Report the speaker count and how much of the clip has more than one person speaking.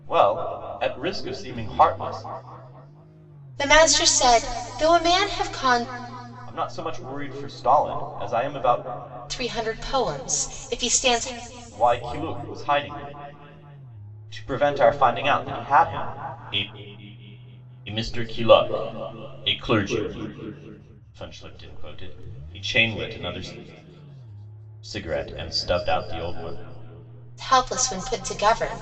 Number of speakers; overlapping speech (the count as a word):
two, no overlap